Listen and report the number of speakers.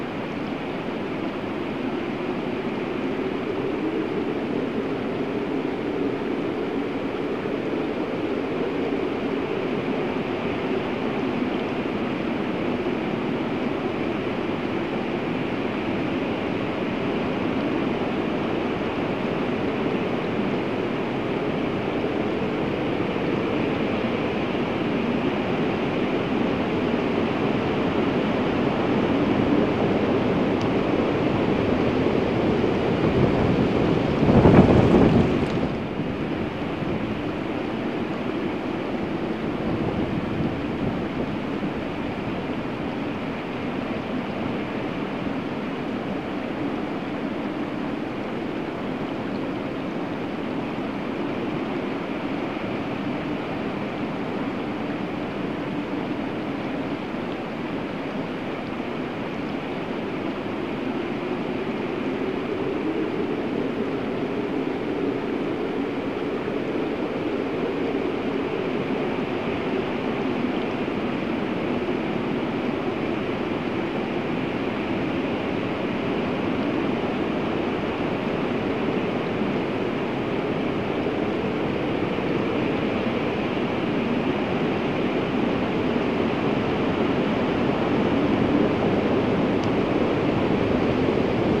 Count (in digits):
0